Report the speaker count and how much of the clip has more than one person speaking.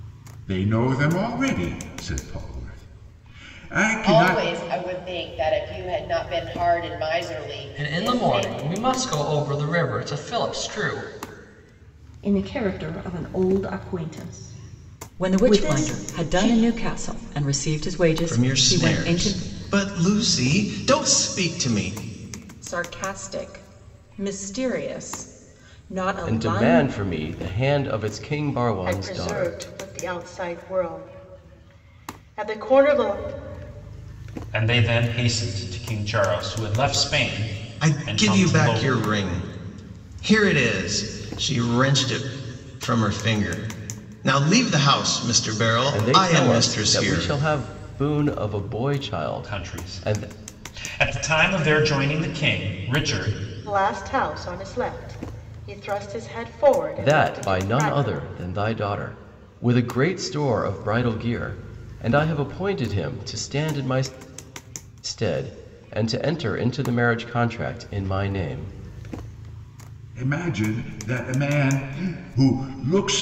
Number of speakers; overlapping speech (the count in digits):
10, about 14%